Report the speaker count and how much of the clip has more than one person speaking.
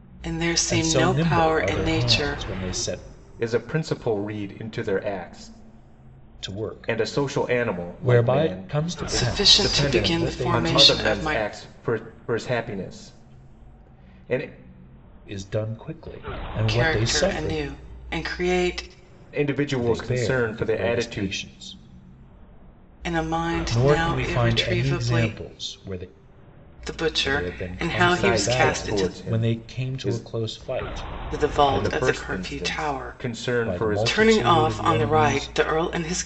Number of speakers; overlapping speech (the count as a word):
three, about 48%